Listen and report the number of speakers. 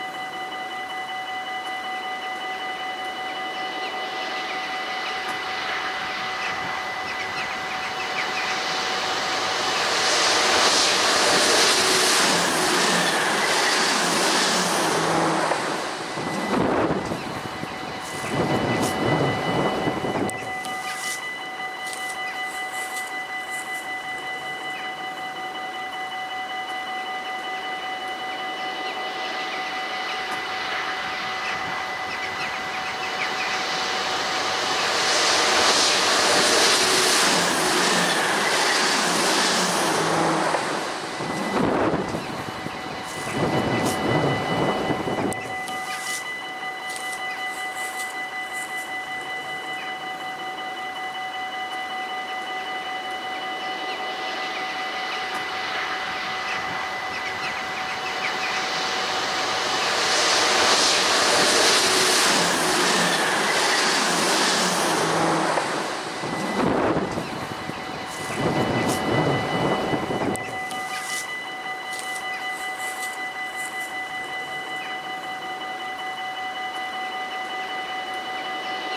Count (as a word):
zero